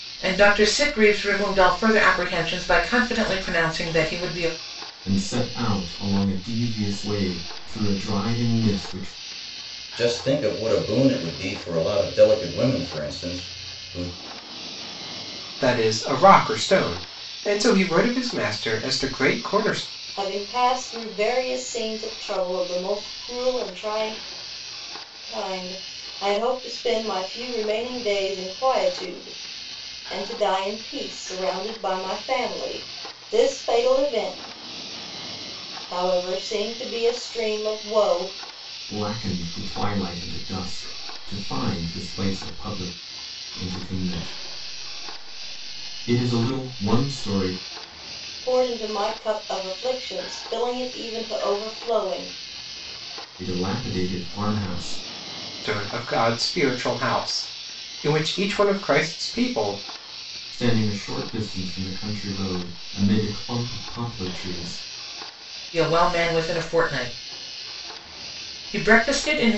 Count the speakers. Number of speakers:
five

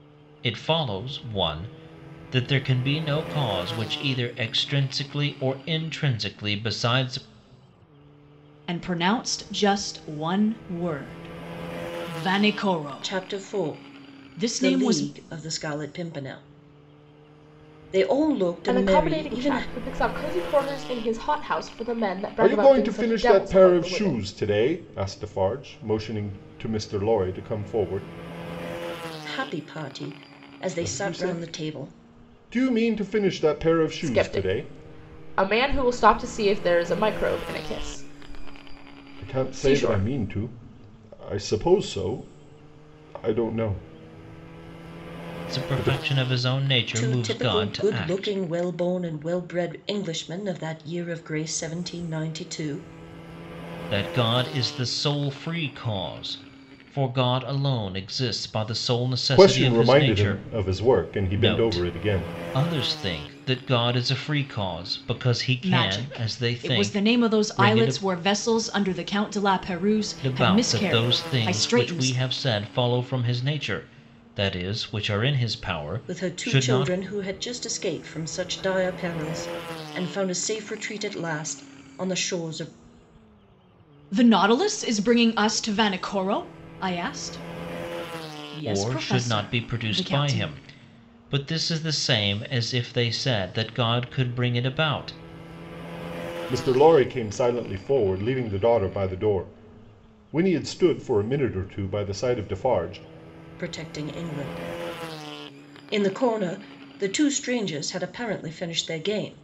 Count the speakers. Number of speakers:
five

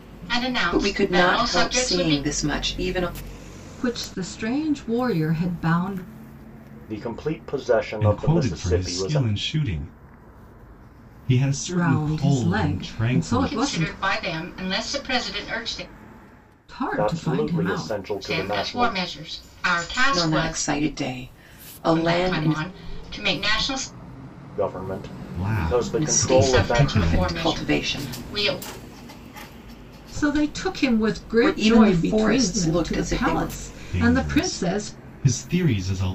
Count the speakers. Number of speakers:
five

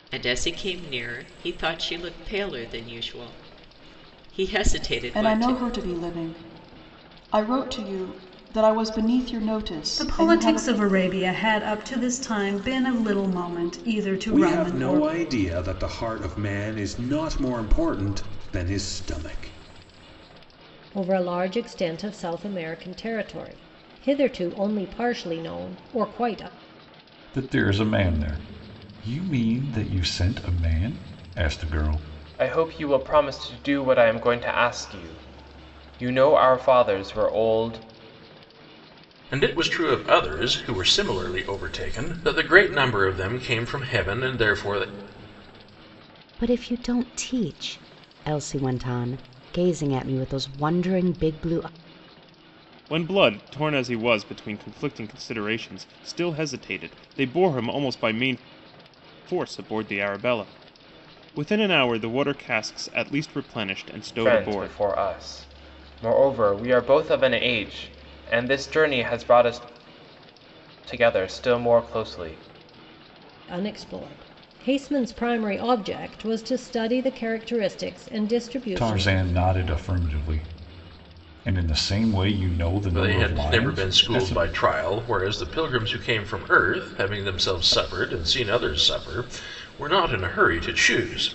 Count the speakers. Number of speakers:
ten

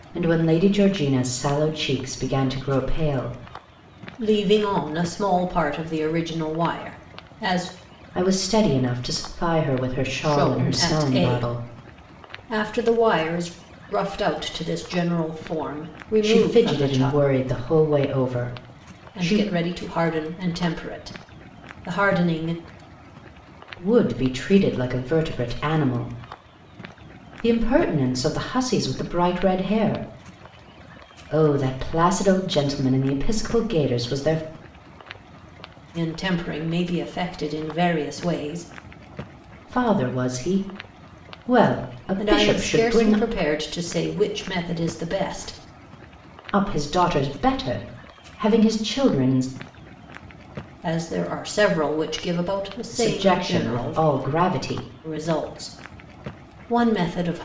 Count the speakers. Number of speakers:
two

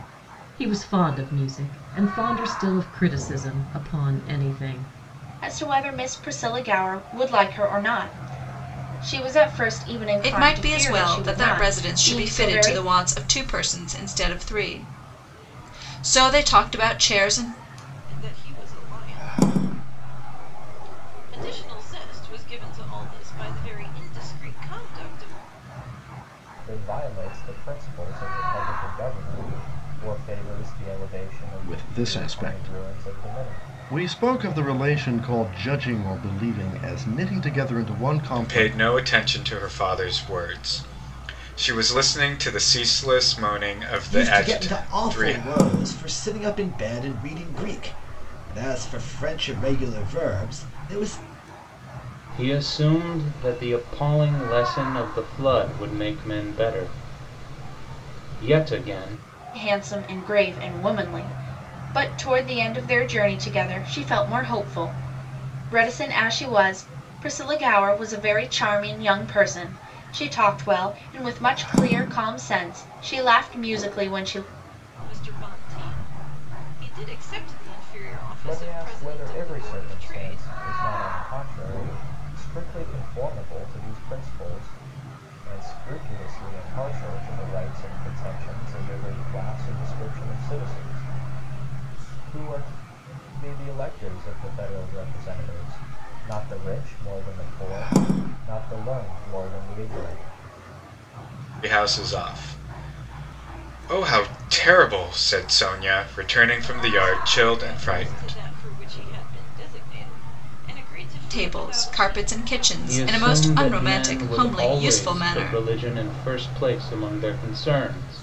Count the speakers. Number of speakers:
nine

